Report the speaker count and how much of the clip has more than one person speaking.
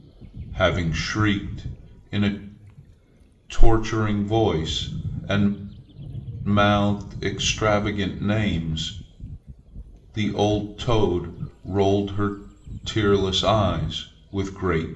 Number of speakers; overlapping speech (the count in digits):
1, no overlap